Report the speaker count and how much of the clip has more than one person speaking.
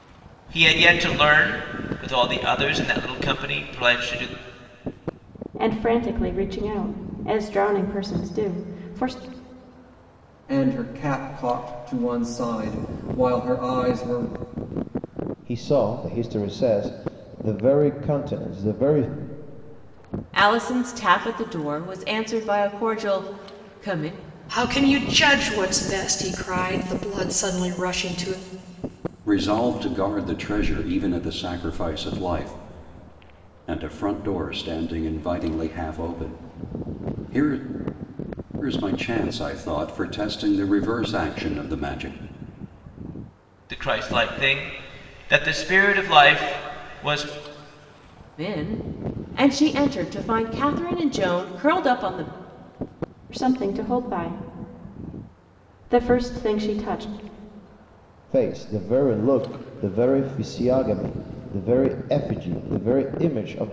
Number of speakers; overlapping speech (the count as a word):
seven, no overlap